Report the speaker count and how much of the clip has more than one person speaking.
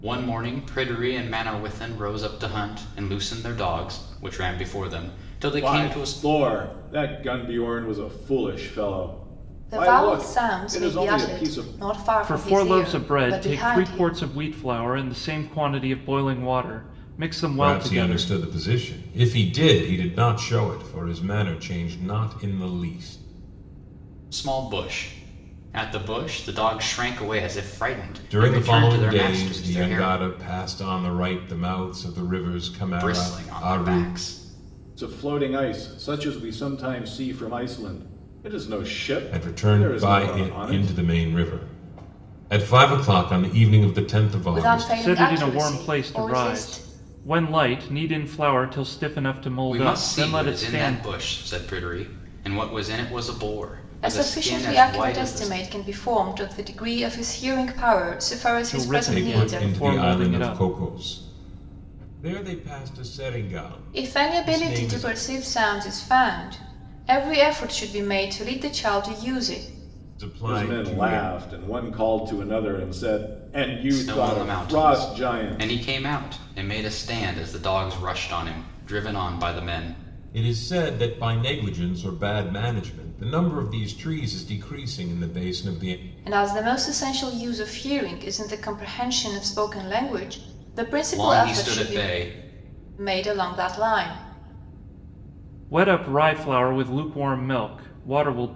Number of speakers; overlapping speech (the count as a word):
five, about 23%